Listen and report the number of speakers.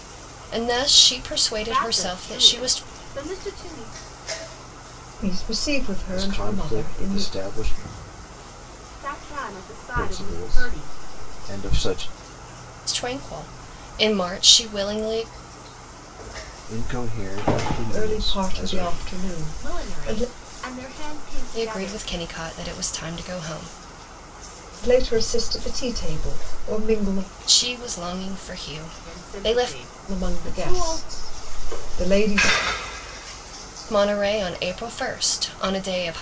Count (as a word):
four